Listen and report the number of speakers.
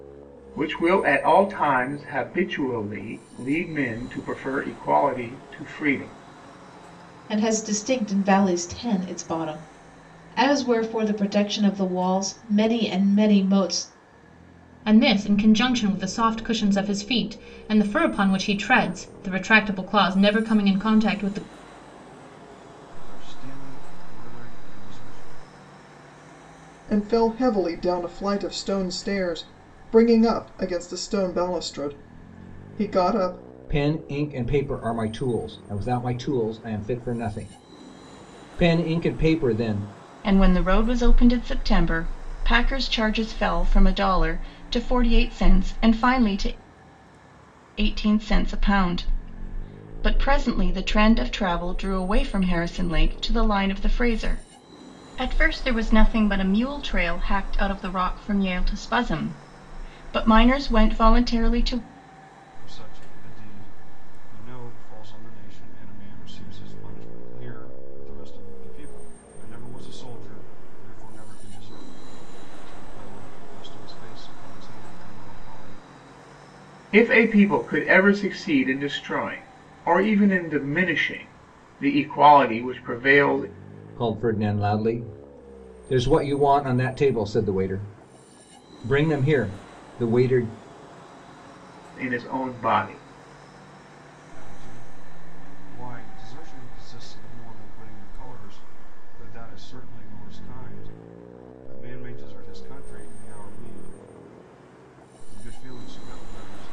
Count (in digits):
7